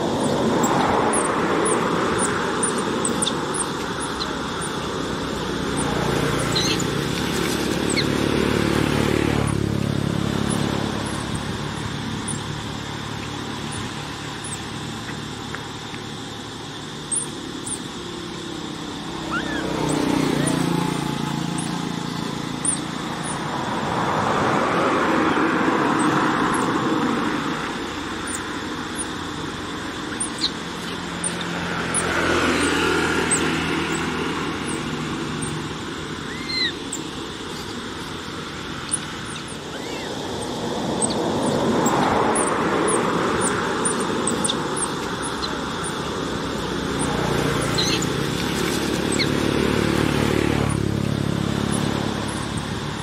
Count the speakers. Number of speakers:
0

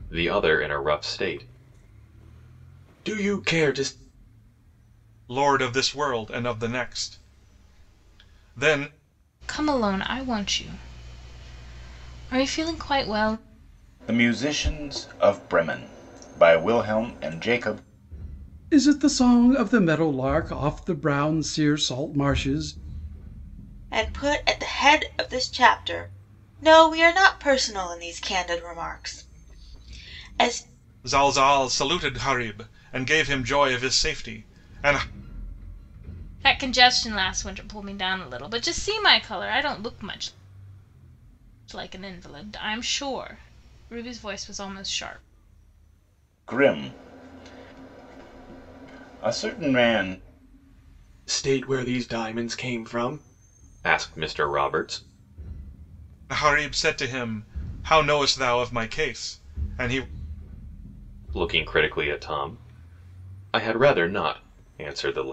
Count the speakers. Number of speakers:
6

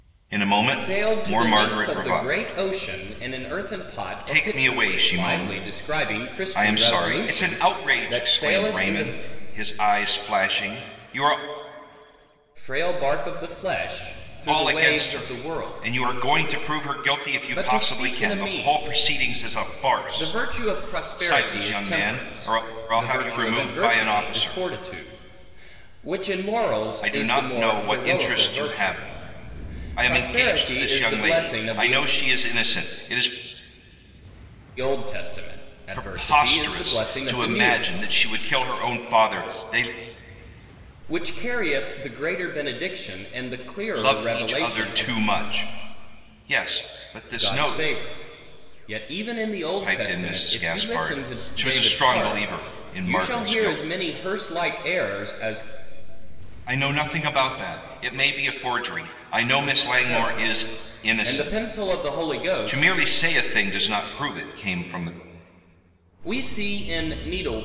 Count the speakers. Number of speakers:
2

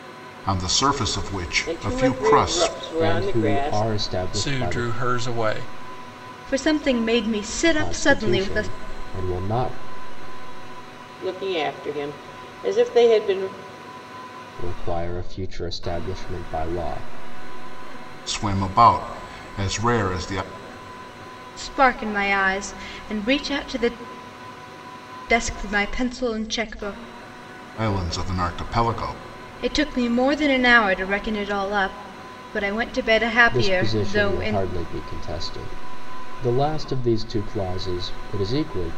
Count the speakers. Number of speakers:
5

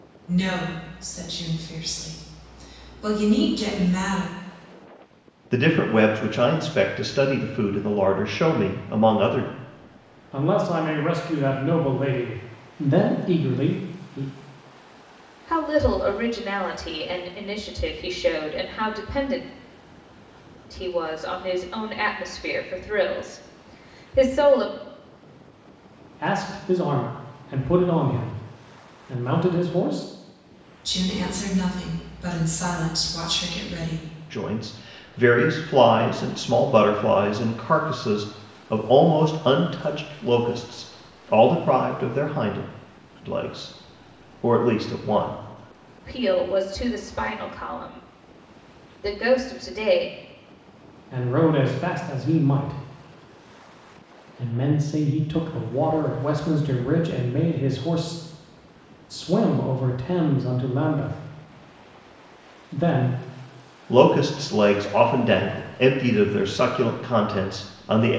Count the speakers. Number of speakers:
4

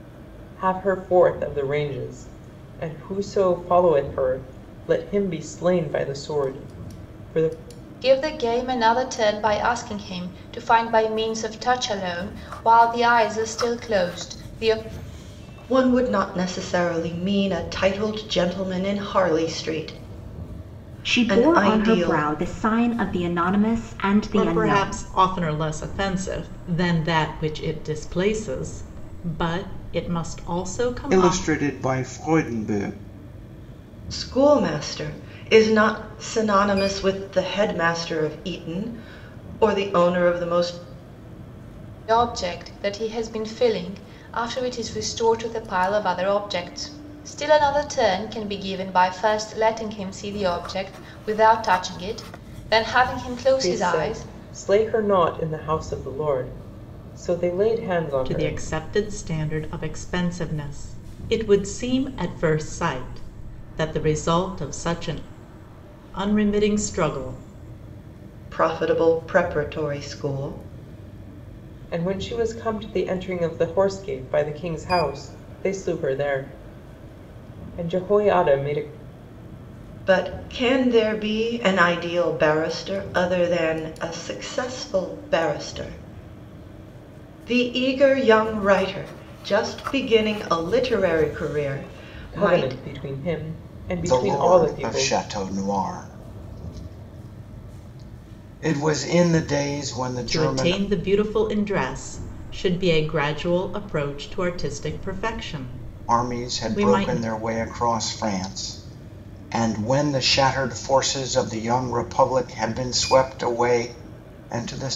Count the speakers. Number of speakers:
6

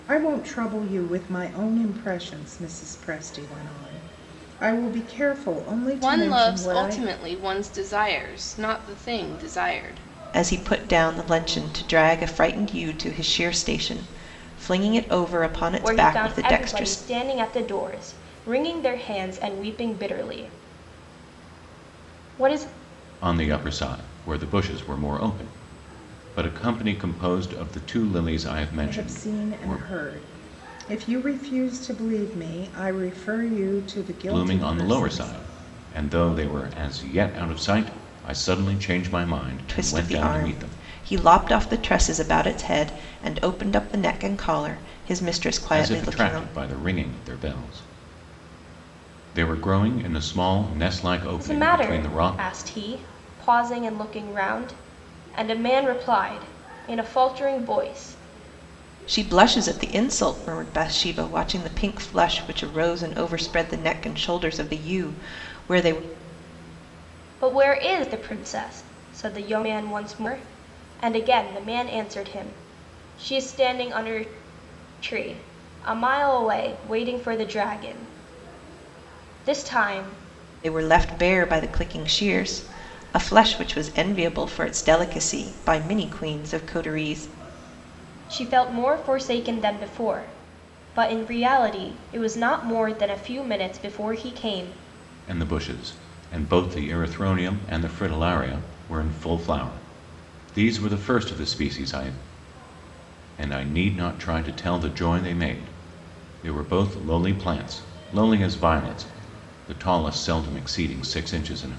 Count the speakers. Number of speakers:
5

